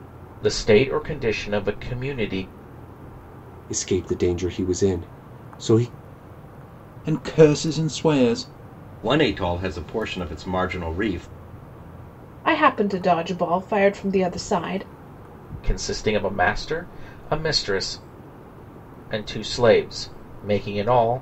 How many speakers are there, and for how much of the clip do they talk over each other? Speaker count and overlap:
five, no overlap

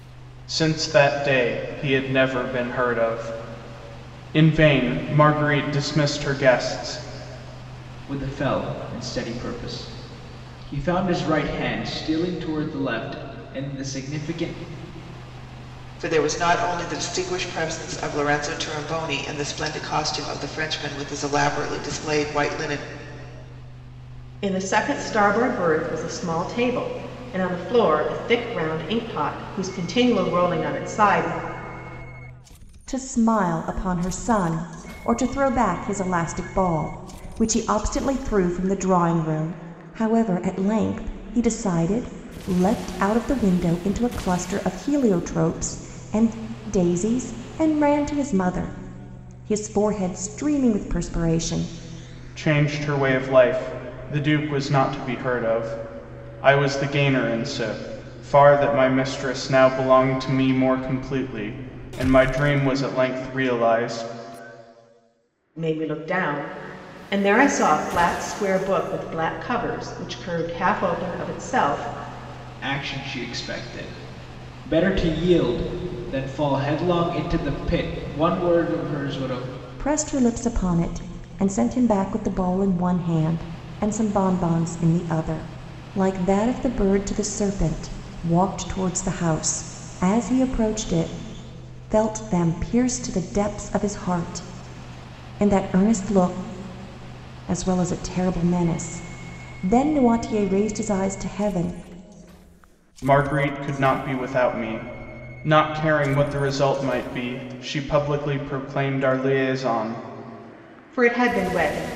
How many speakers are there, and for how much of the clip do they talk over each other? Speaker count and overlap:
five, no overlap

